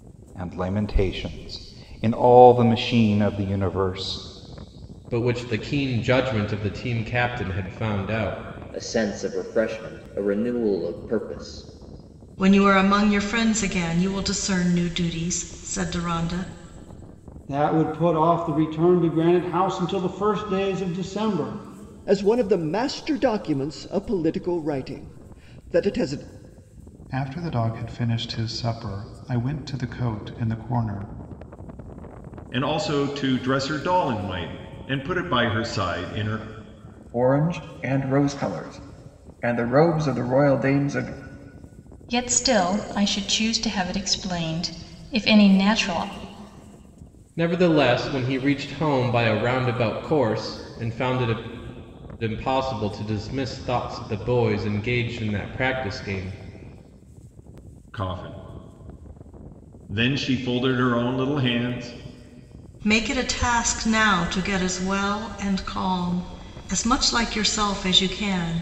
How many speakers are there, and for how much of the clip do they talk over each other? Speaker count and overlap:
ten, no overlap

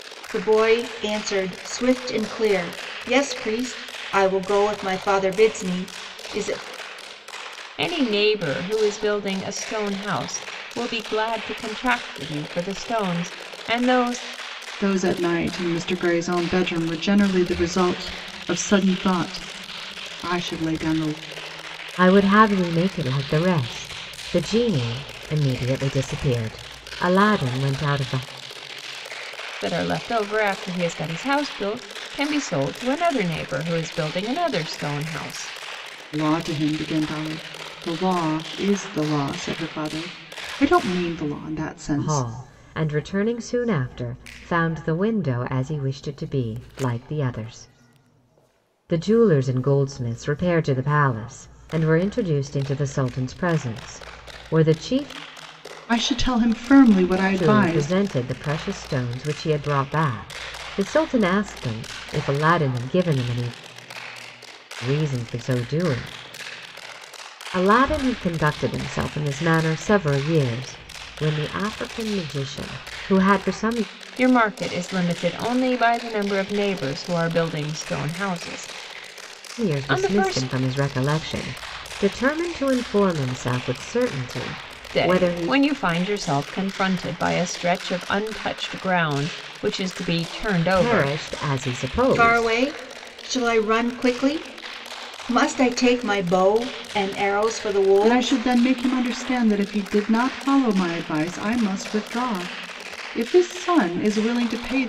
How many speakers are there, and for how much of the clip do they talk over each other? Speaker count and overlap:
four, about 4%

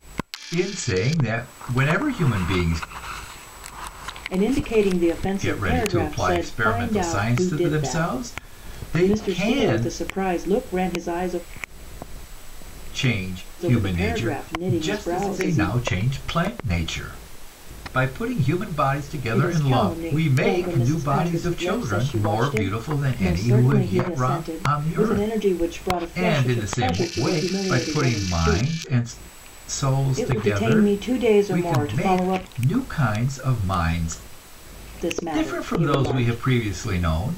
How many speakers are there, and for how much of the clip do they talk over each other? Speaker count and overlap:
two, about 50%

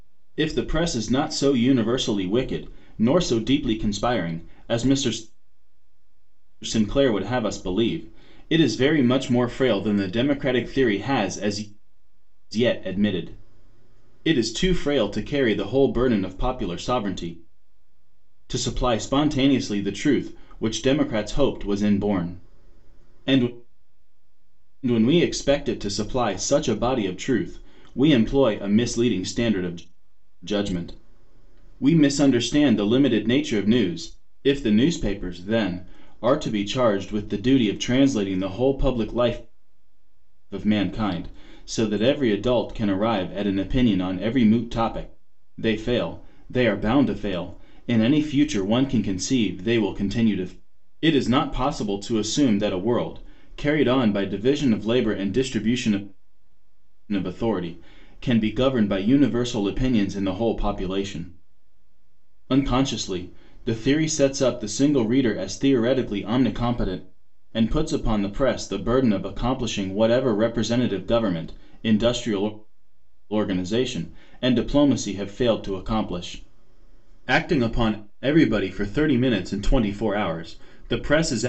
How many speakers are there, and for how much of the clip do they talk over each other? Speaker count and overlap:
one, no overlap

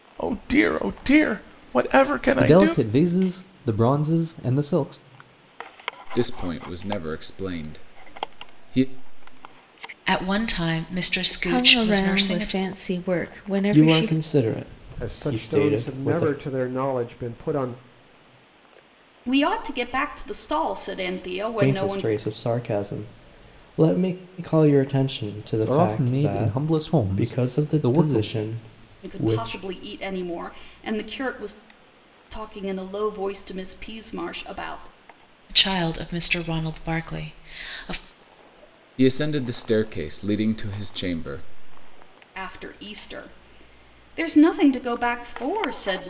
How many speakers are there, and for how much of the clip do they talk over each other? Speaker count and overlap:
eight, about 15%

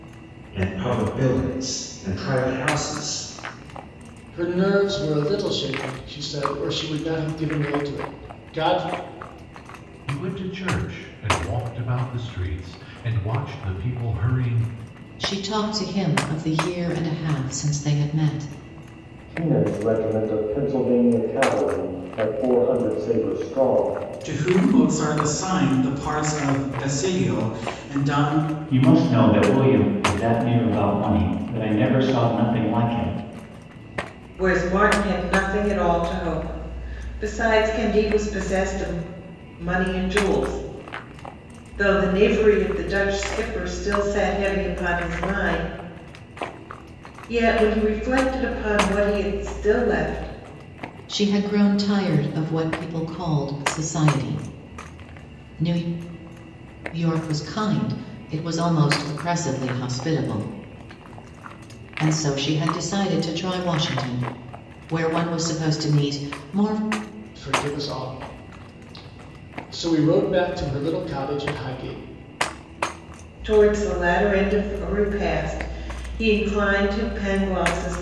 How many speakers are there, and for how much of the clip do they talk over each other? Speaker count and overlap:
eight, no overlap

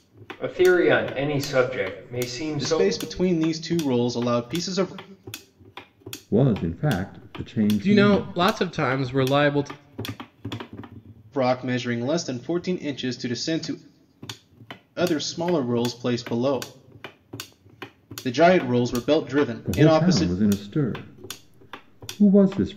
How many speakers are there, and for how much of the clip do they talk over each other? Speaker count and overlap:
four, about 8%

